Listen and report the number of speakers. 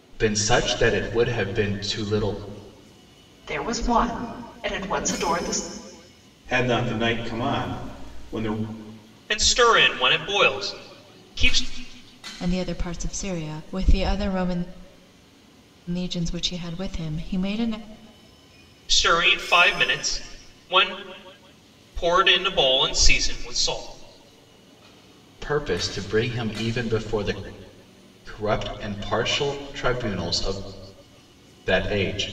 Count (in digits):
5